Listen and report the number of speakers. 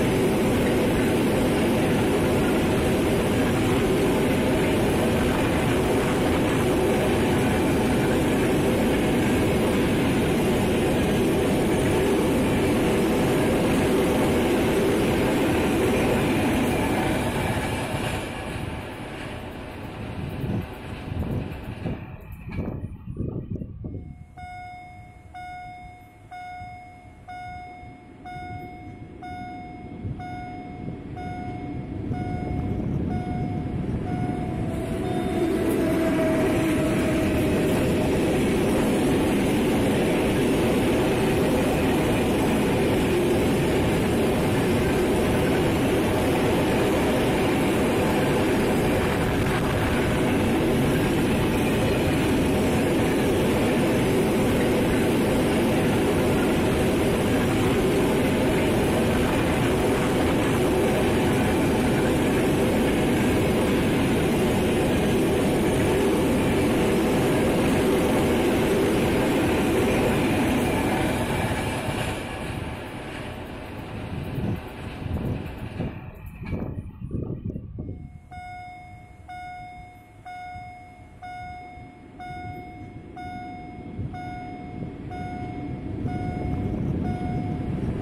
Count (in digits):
0